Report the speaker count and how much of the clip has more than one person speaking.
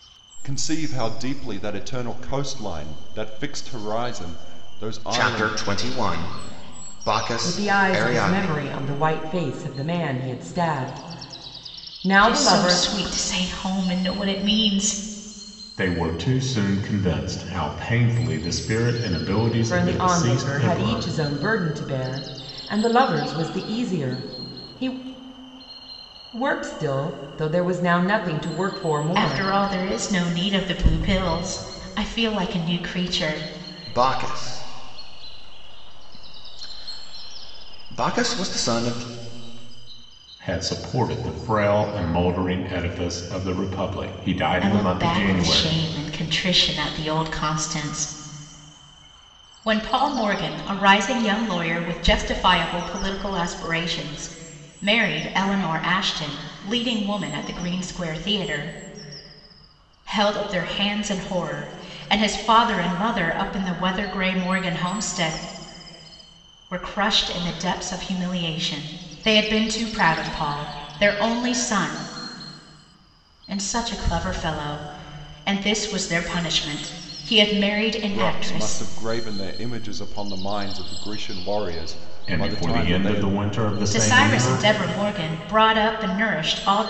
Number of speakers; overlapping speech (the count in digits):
5, about 9%